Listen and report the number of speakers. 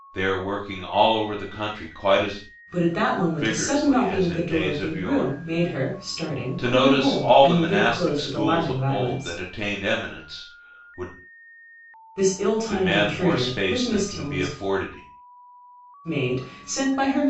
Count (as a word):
two